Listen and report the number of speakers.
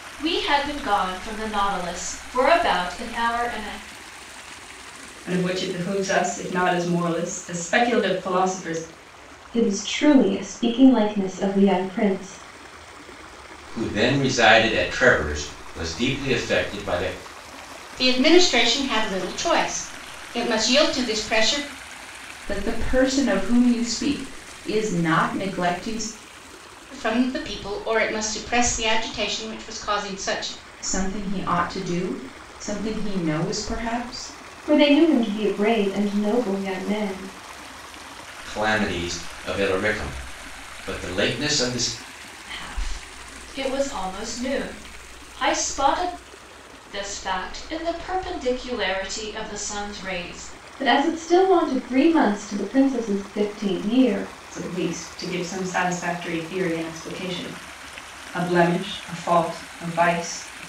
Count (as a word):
six